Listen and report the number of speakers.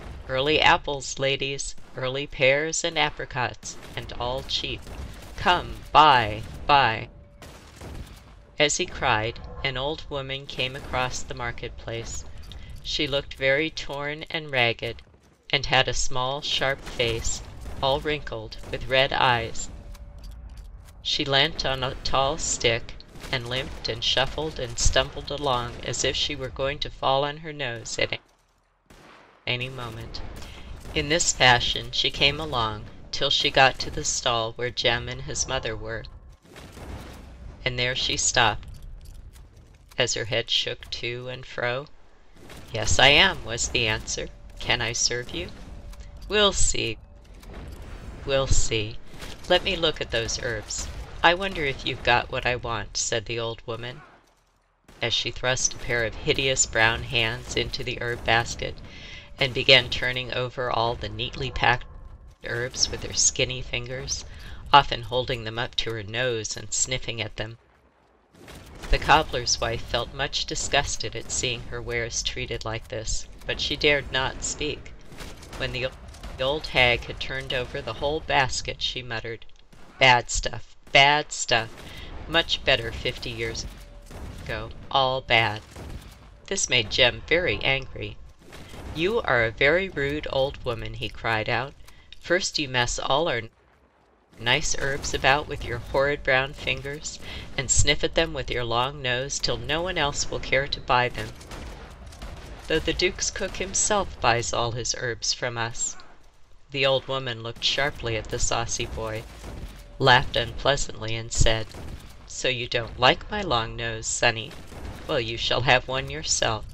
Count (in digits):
1